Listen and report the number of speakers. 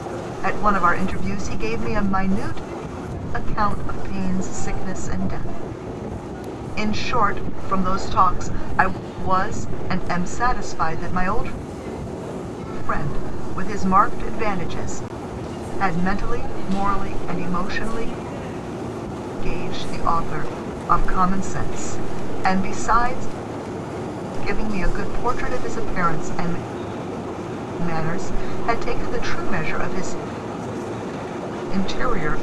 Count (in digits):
1